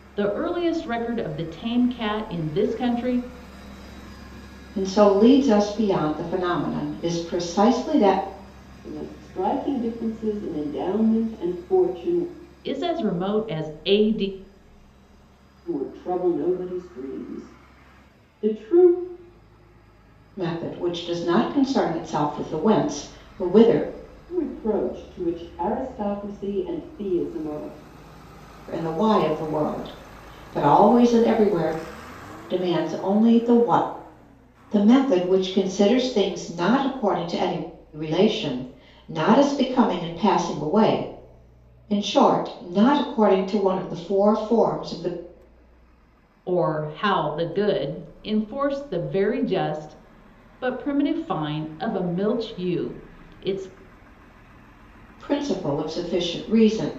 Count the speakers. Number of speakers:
three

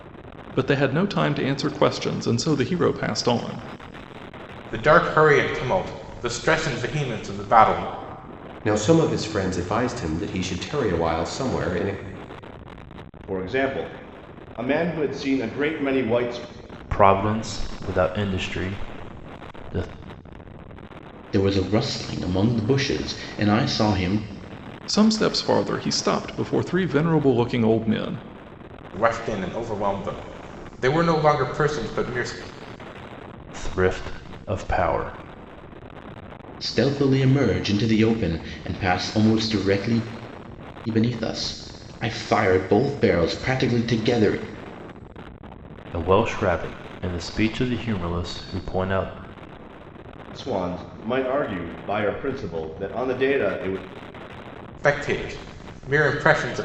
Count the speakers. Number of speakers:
six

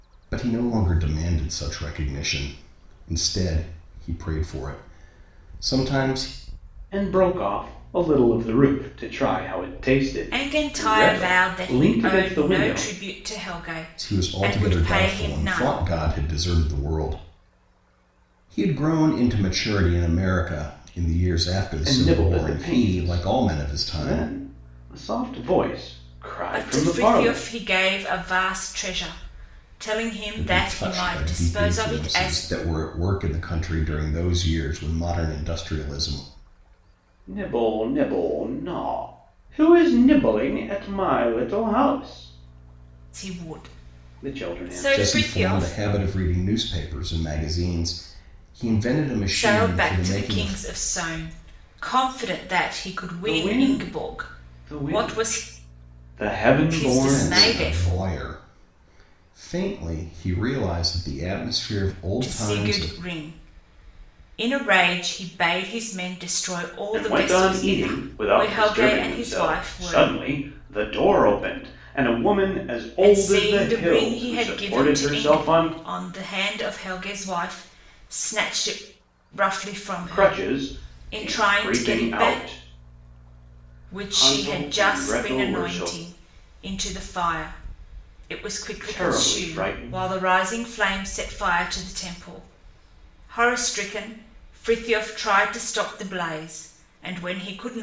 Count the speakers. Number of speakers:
three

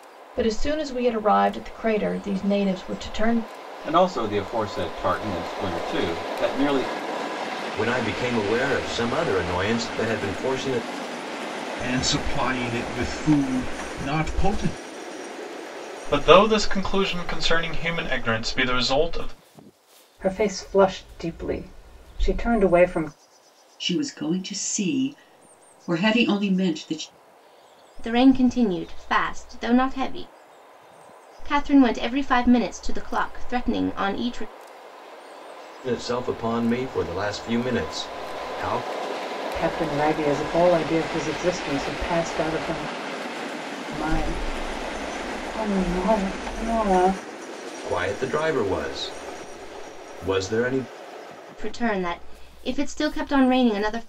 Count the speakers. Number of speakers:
eight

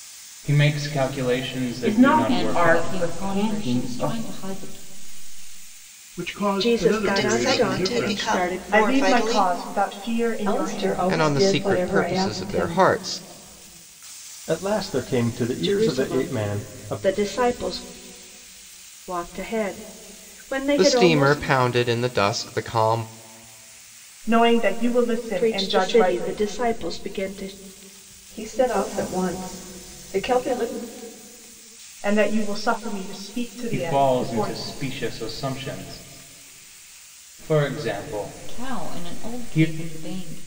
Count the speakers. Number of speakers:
ten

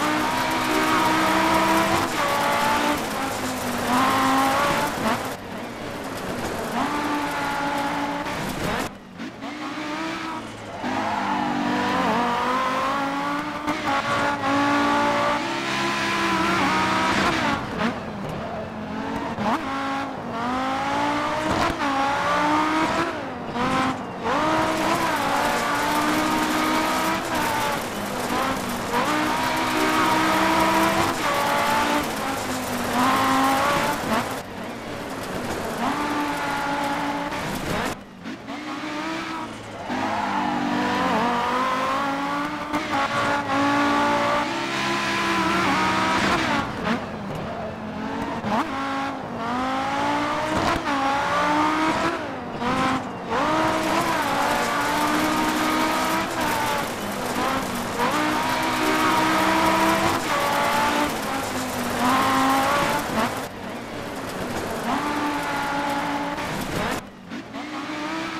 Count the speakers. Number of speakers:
zero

